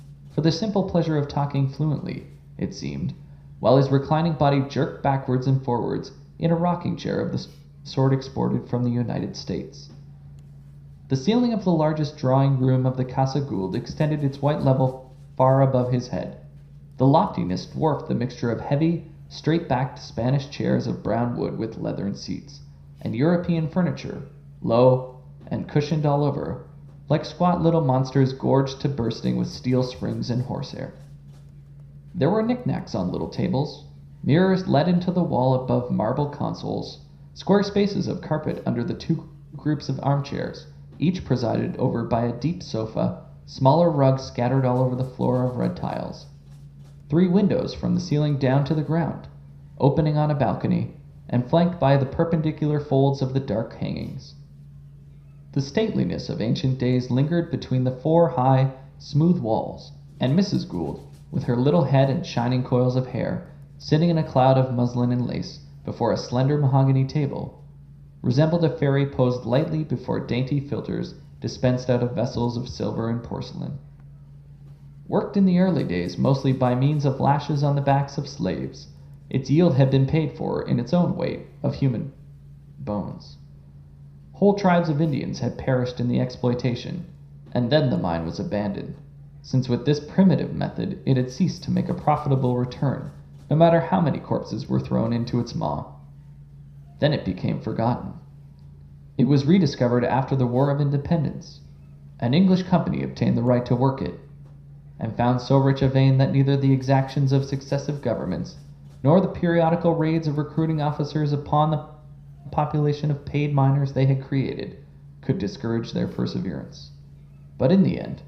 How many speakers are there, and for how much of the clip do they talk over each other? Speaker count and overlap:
1, no overlap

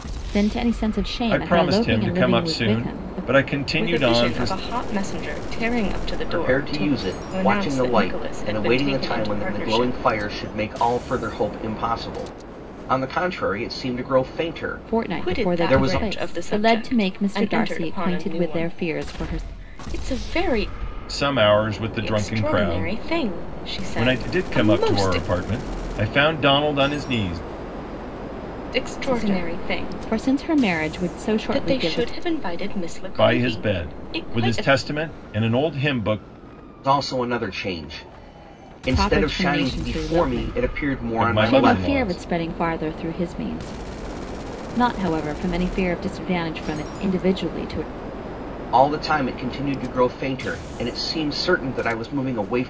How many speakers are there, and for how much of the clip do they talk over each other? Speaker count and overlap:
4, about 38%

